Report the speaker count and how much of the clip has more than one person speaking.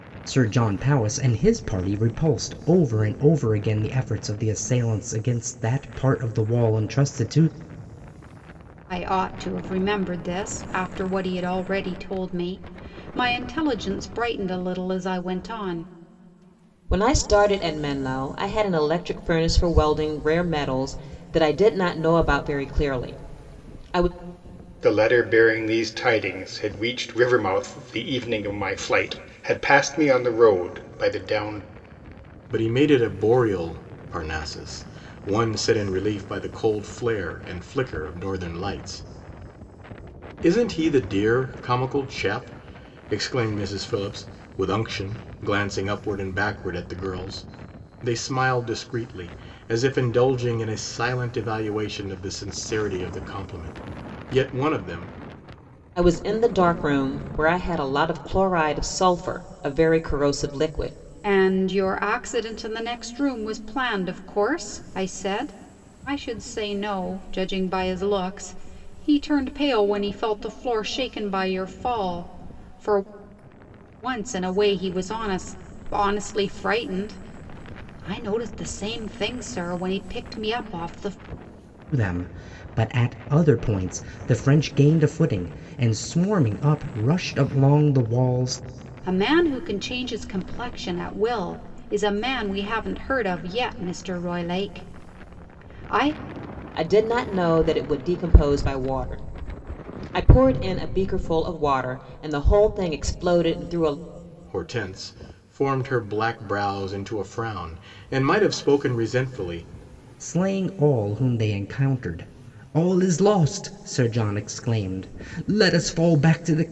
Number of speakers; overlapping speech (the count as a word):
five, no overlap